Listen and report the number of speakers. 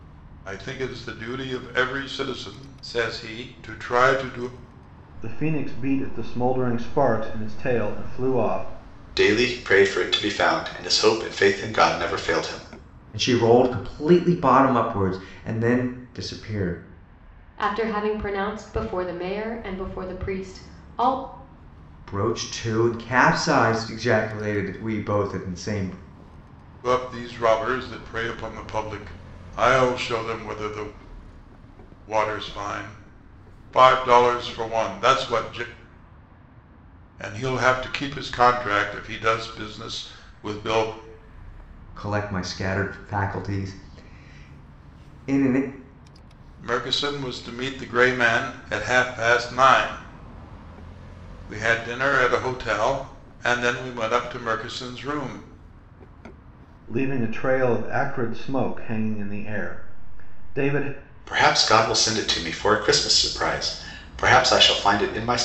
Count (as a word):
five